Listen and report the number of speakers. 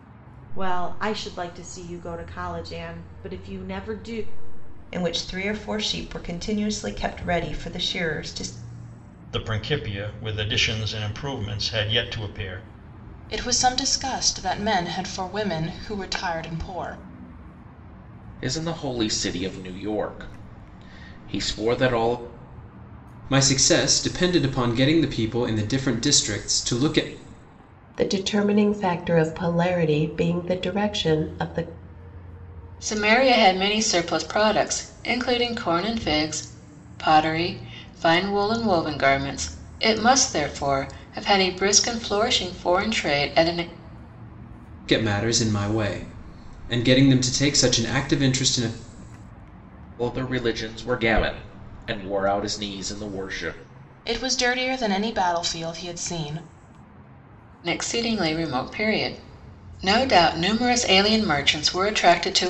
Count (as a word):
eight